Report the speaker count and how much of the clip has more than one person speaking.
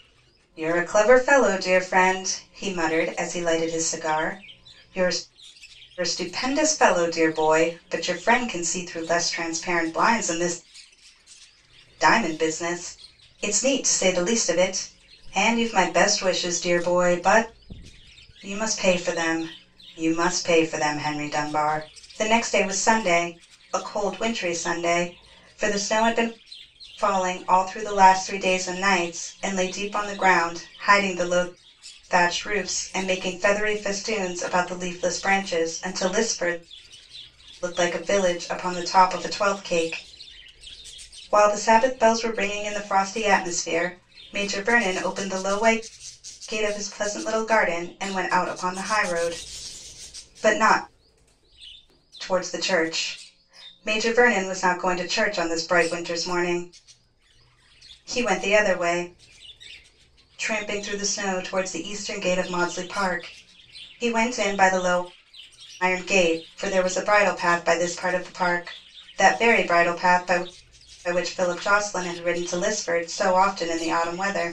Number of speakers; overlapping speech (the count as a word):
one, no overlap